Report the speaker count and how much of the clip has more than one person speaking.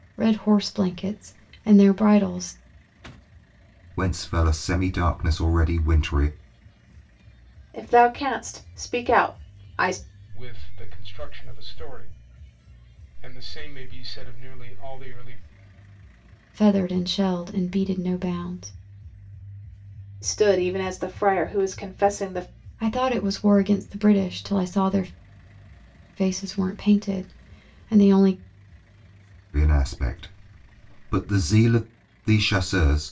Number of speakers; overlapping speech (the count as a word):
four, no overlap